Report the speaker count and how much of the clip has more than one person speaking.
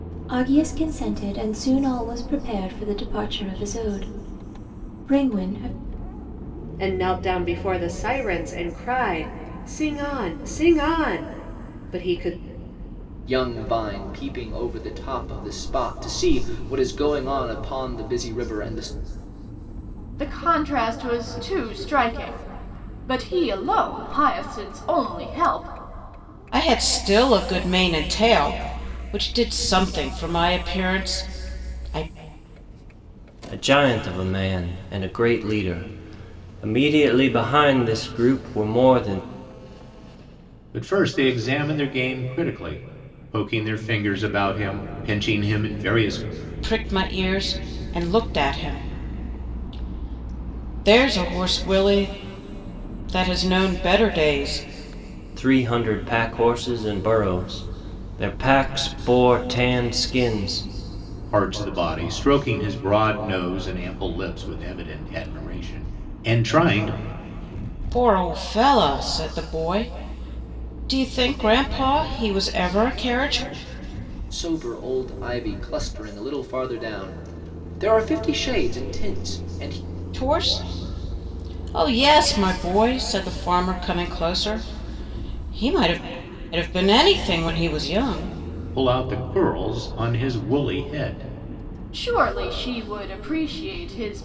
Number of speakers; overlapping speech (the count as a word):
seven, no overlap